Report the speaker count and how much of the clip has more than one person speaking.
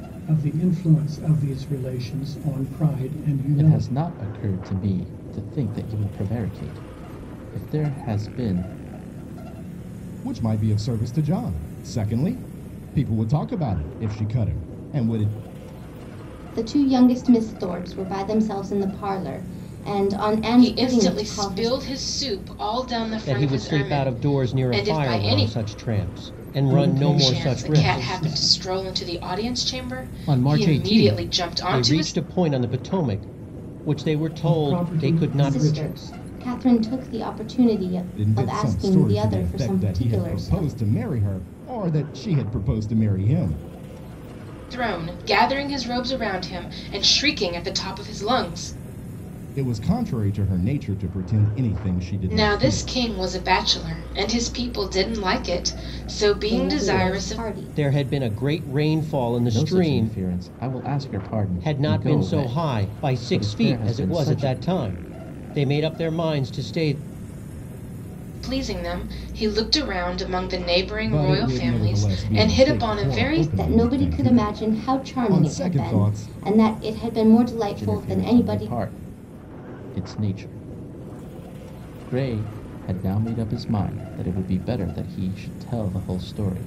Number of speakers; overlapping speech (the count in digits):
6, about 28%